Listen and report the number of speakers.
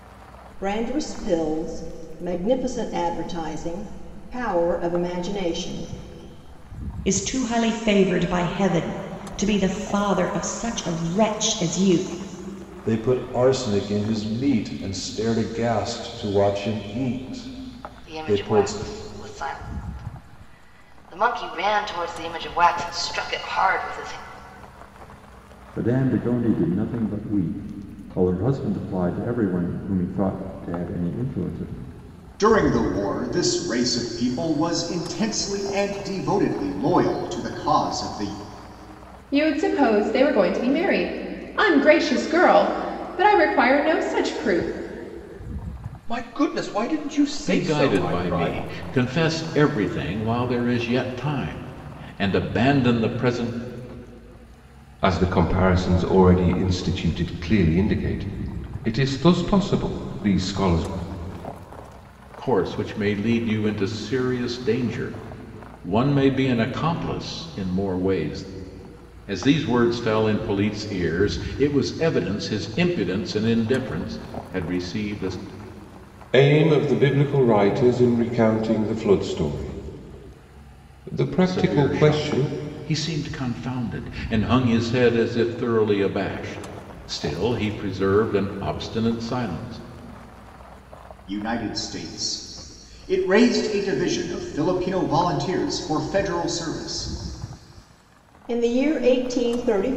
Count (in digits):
10